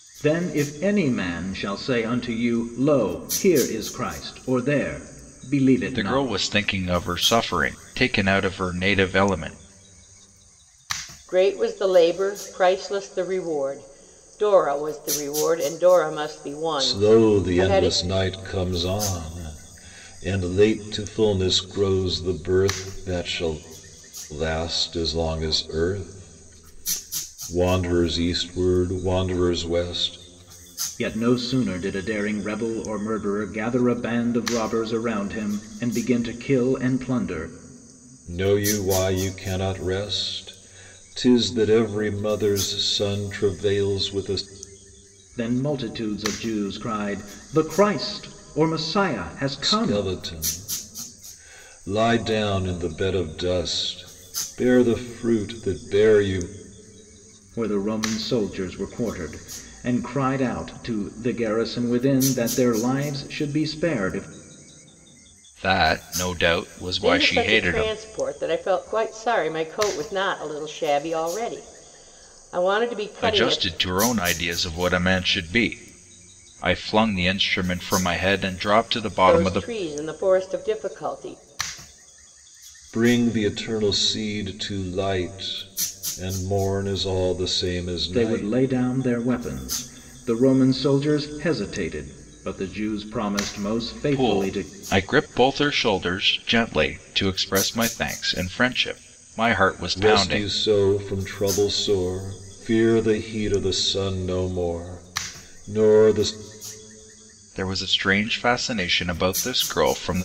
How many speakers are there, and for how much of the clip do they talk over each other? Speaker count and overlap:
4, about 5%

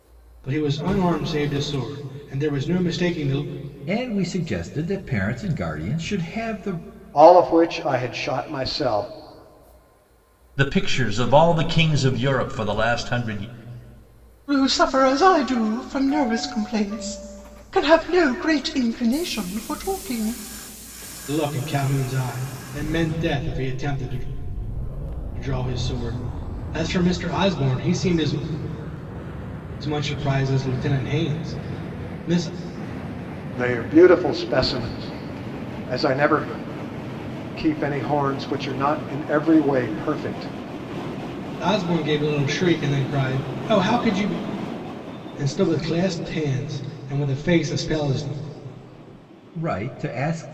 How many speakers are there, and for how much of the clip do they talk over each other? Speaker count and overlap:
5, no overlap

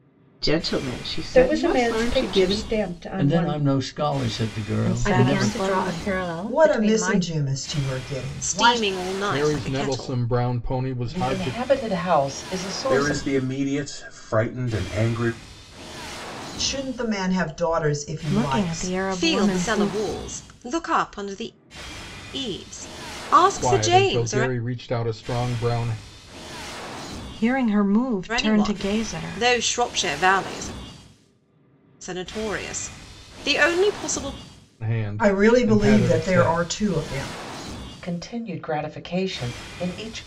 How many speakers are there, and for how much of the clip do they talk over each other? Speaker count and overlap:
10, about 29%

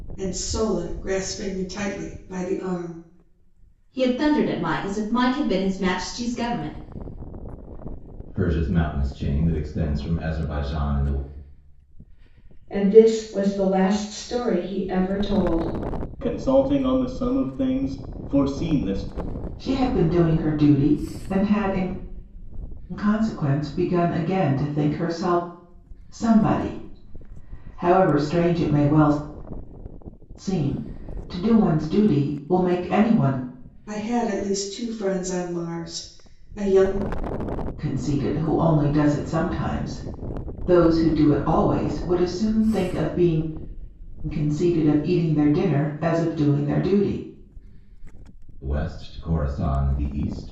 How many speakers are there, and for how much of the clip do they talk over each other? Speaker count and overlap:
6, no overlap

